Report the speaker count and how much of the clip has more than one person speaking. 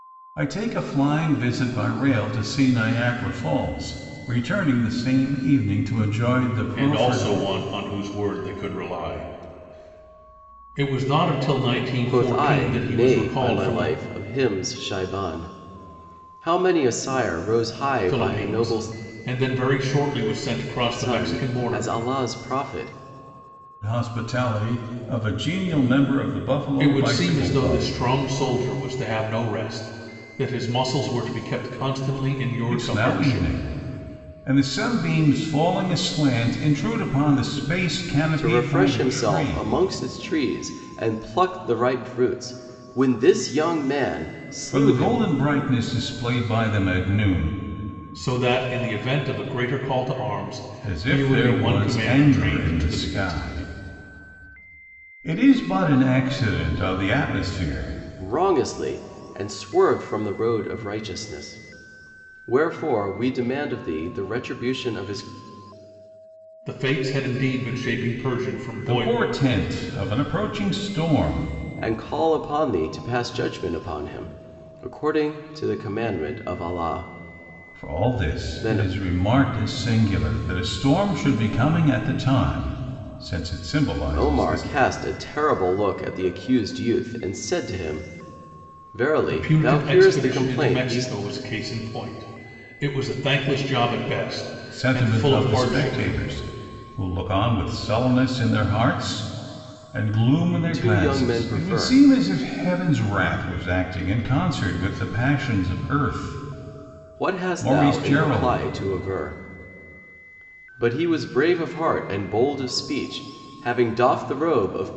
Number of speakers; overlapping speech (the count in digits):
3, about 17%